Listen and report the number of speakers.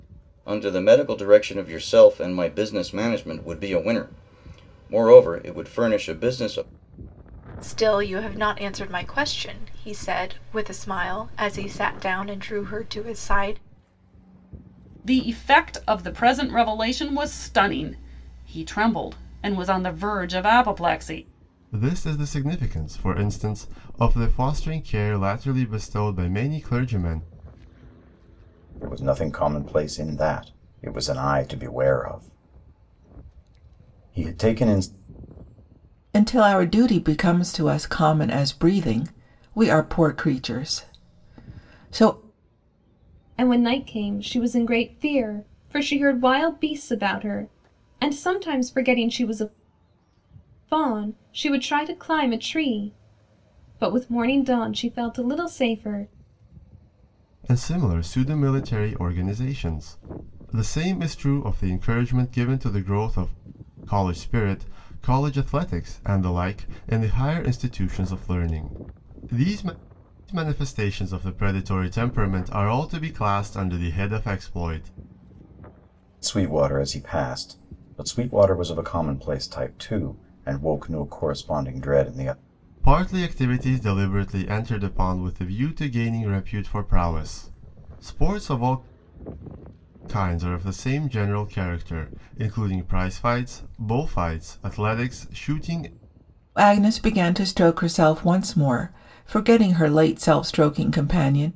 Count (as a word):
seven